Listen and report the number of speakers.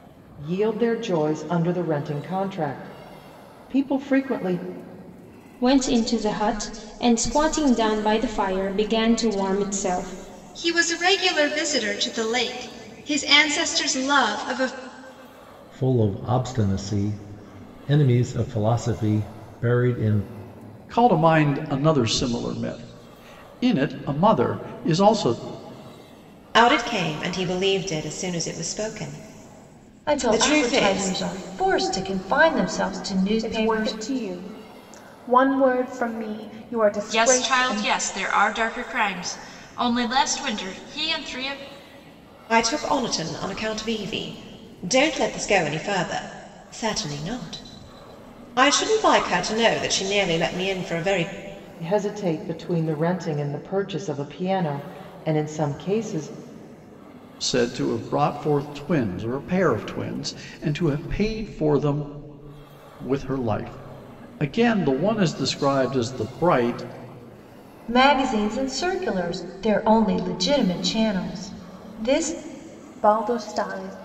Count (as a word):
nine